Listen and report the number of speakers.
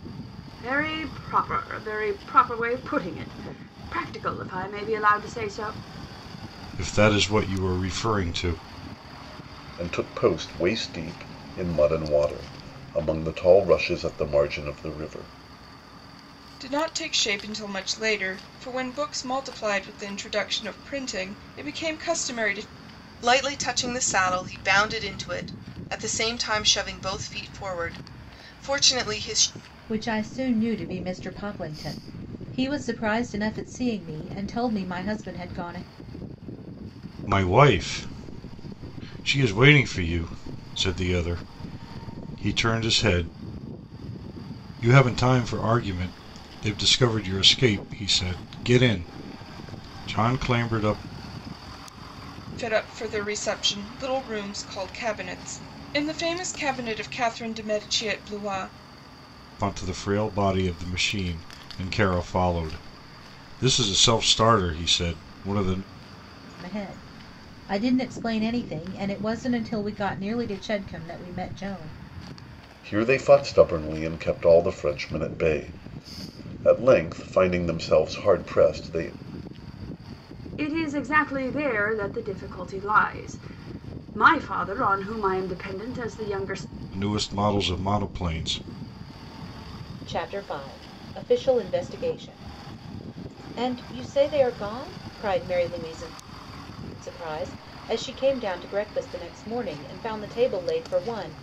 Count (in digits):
6